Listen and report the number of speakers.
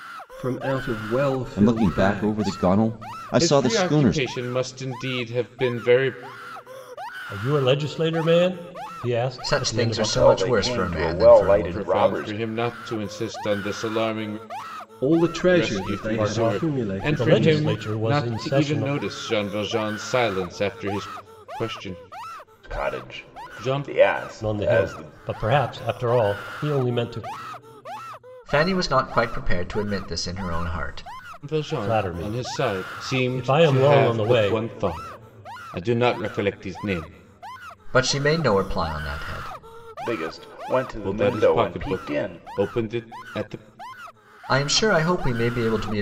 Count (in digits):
6